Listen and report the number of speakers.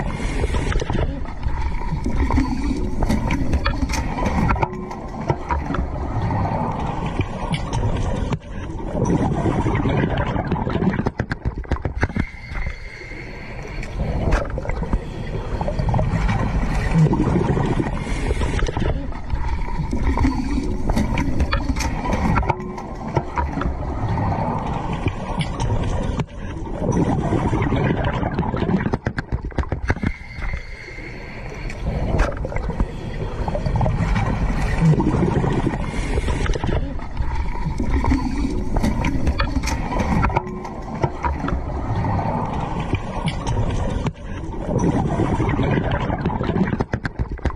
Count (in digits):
0